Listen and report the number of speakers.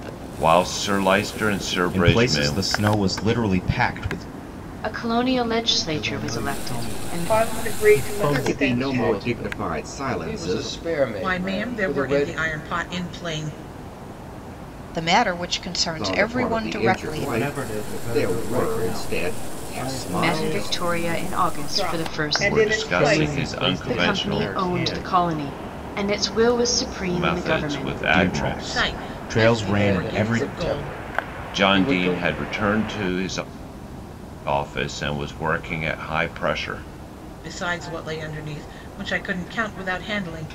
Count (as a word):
ten